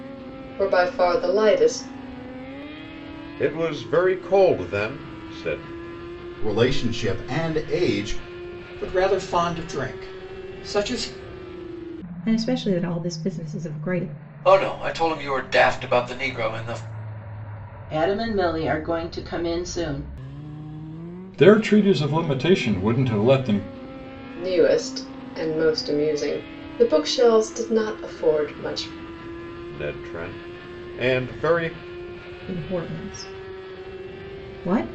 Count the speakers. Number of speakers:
eight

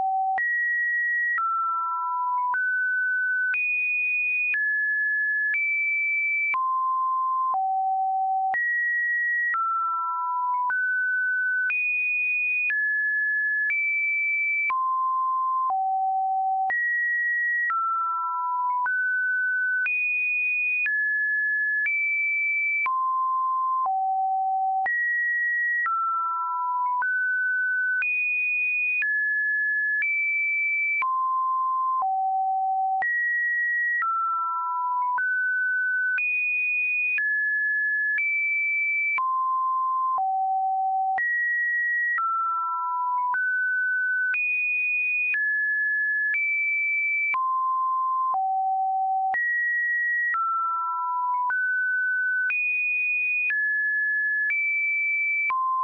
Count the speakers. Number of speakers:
zero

